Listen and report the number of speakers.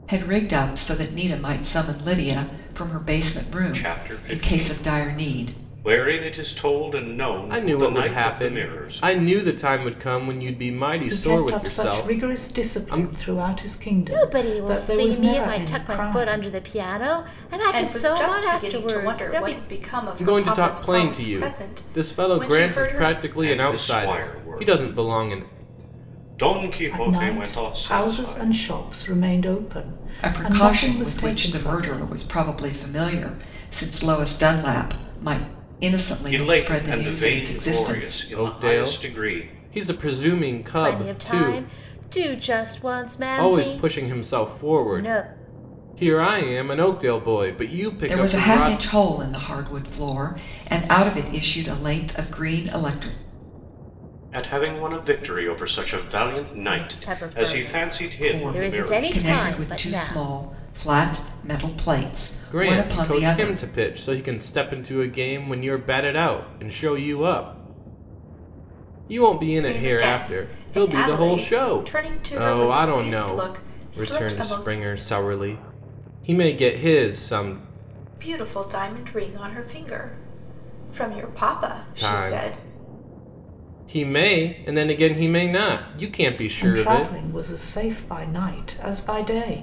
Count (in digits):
6